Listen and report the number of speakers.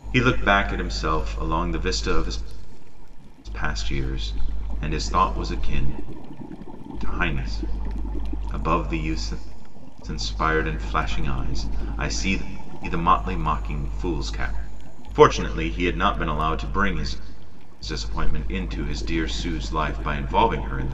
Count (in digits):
1